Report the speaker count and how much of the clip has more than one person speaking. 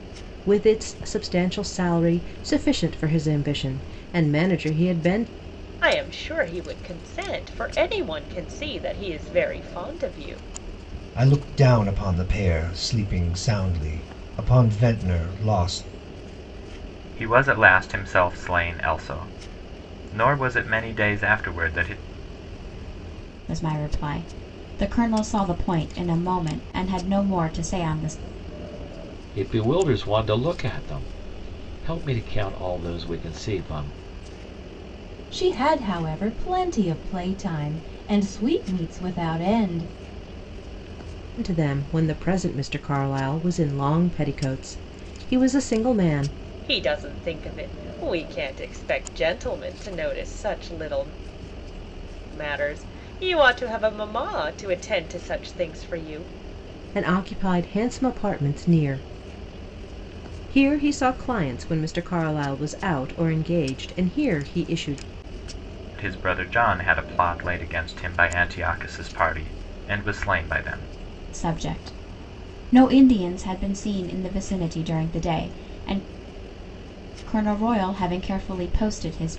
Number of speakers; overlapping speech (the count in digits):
7, no overlap